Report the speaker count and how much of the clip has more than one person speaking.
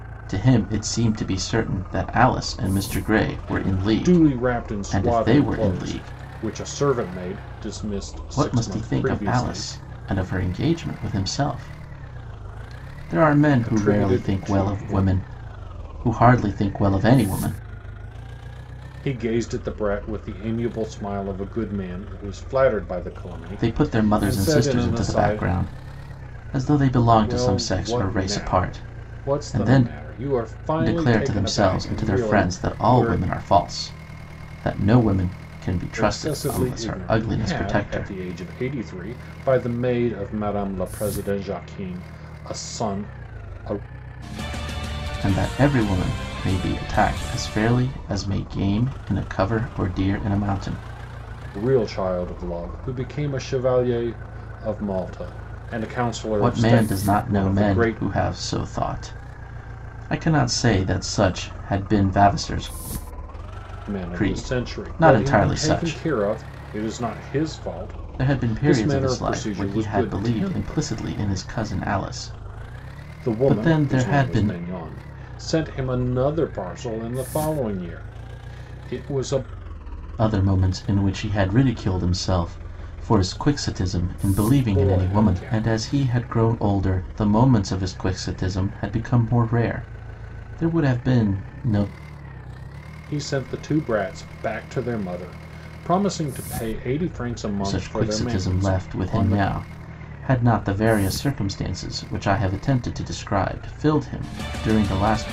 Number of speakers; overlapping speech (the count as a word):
two, about 25%